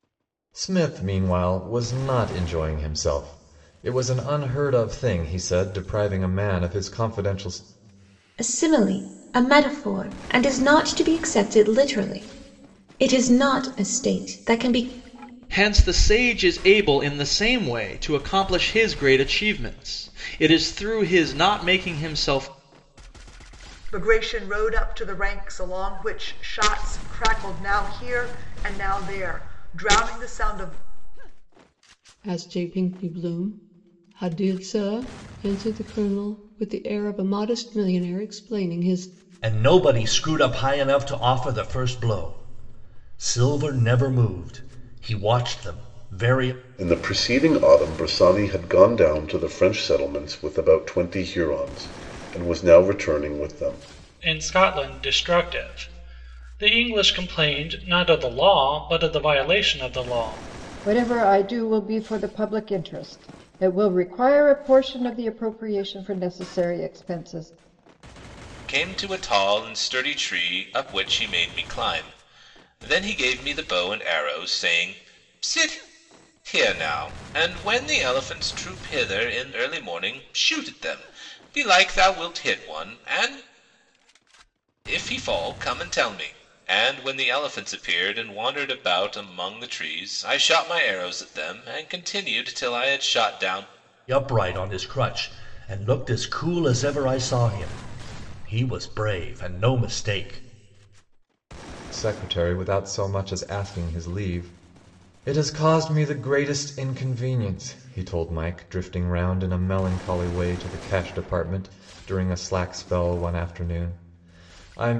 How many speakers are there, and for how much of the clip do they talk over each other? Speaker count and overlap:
ten, no overlap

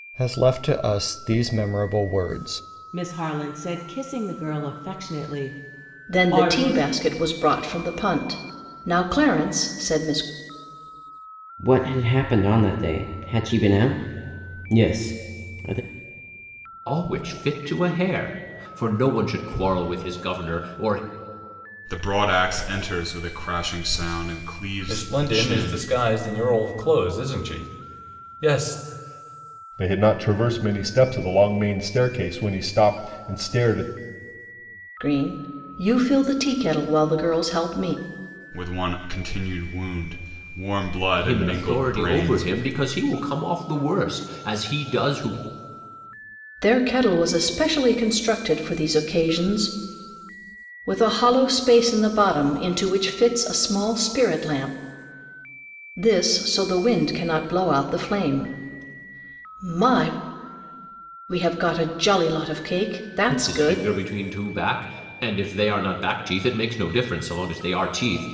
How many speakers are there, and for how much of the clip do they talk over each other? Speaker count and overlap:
eight, about 6%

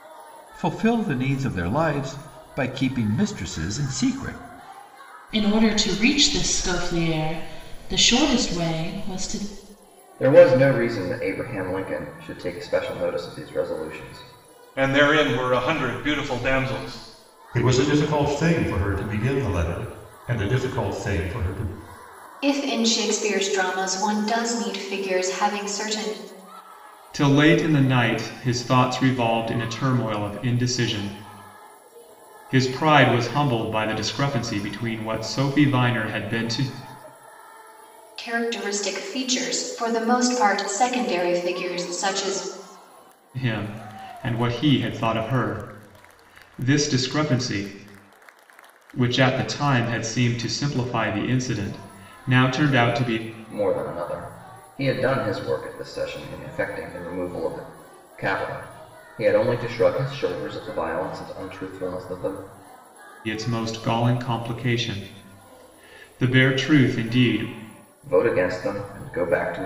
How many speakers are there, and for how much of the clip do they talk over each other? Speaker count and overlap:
seven, no overlap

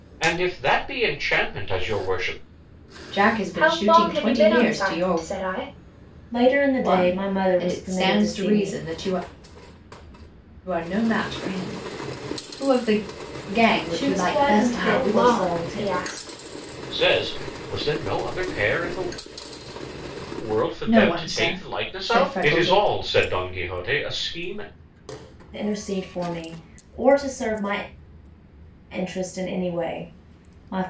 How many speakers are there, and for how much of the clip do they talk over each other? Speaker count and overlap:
four, about 24%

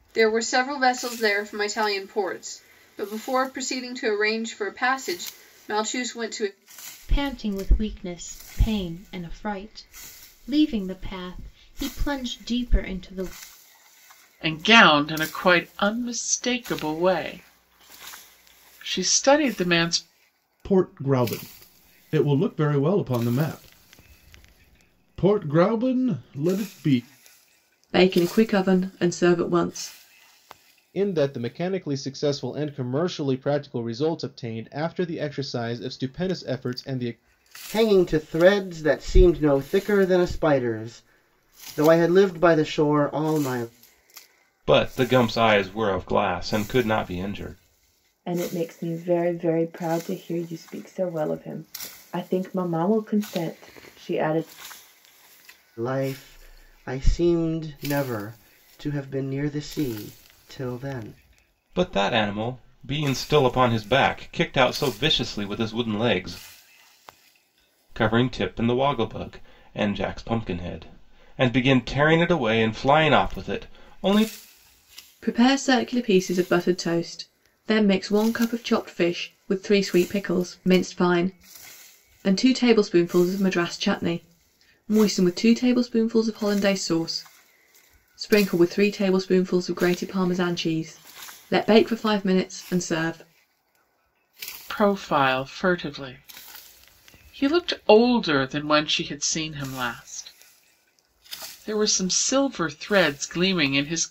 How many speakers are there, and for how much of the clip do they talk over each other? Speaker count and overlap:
nine, no overlap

